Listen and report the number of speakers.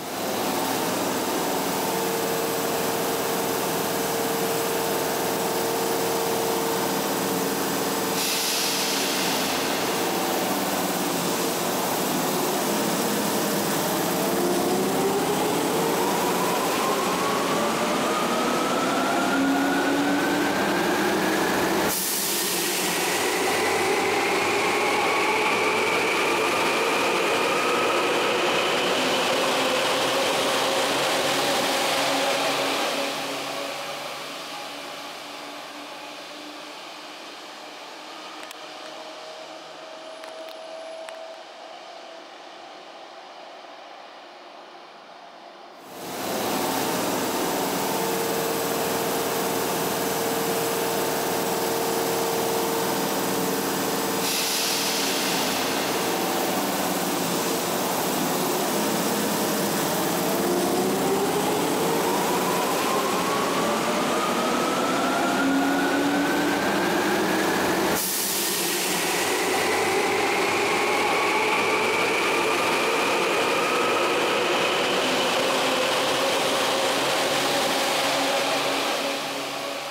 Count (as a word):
zero